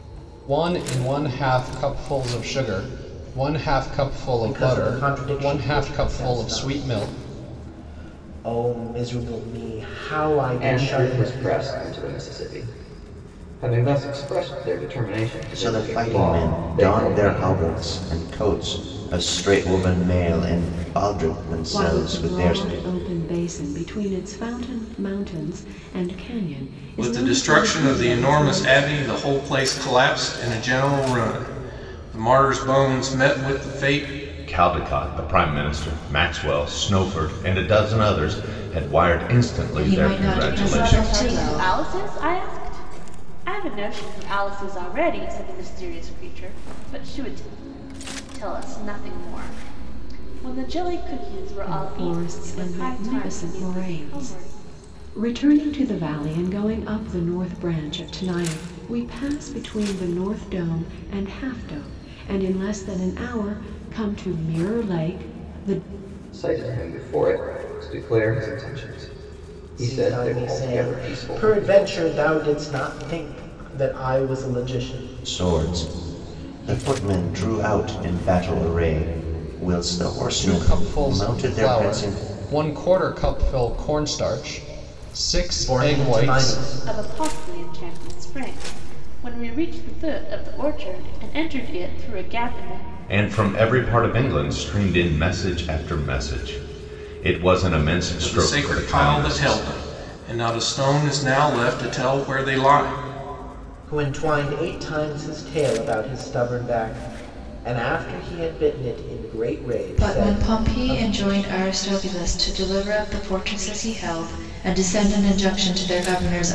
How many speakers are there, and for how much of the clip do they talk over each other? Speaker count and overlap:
9, about 20%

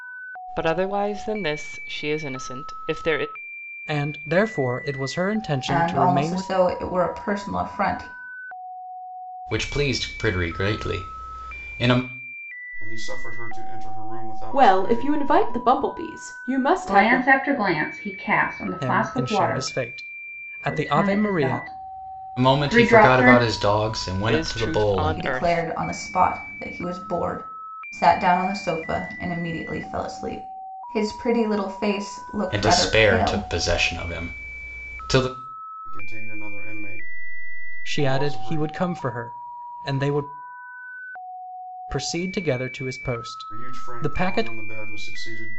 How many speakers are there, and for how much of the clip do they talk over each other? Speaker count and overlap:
7, about 21%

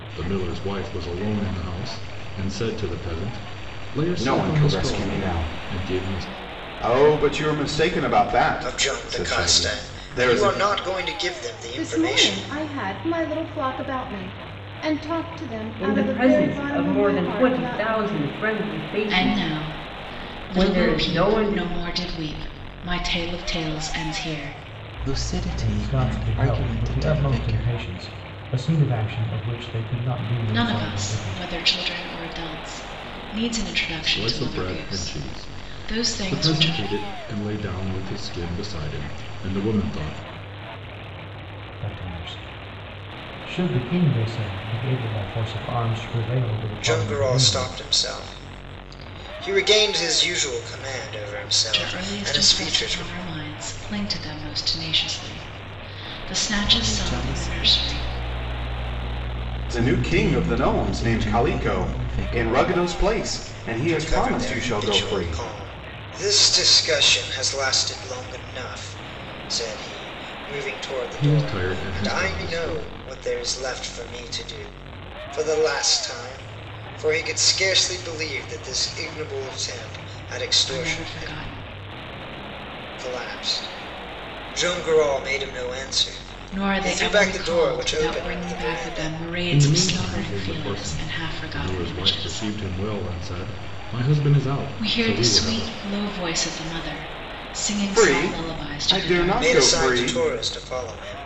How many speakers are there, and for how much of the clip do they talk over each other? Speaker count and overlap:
8, about 34%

